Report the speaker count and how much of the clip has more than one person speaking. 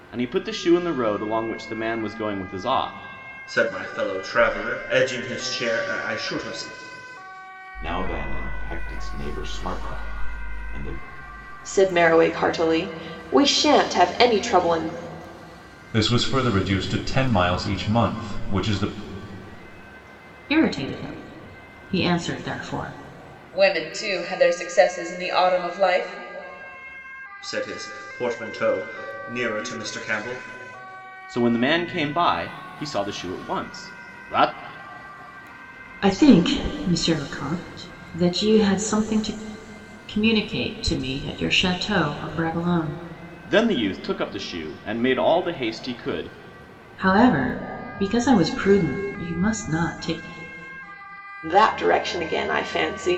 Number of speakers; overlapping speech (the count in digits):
7, no overlap